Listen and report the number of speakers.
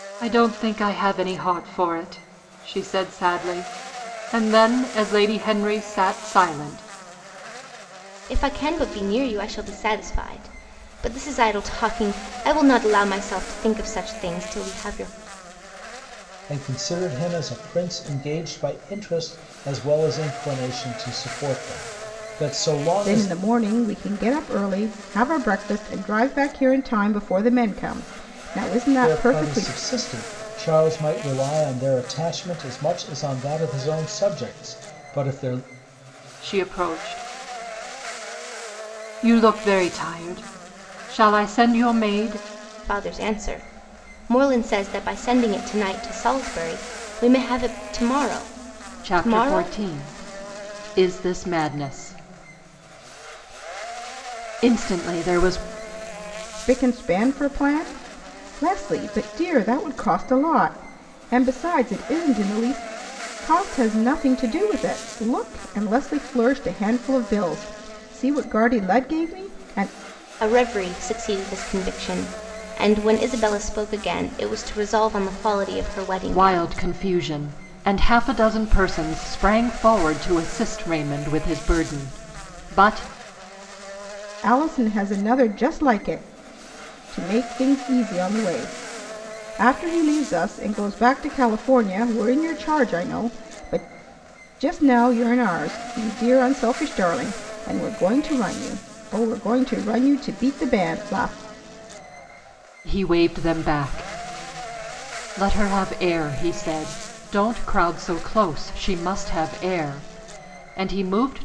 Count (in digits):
4